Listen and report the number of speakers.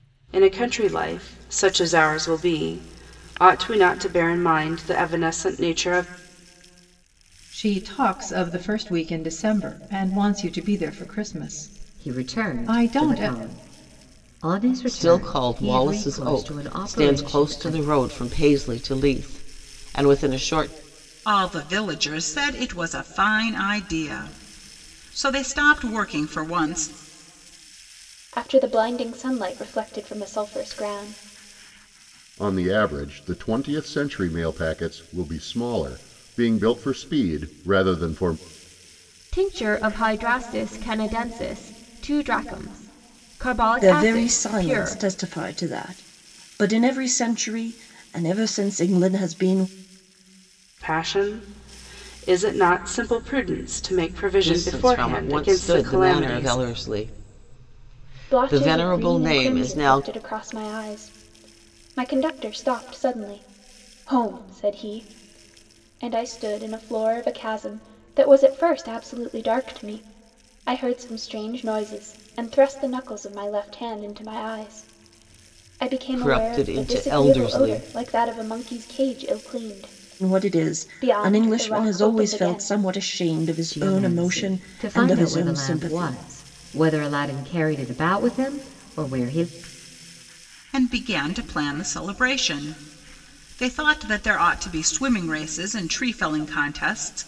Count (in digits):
9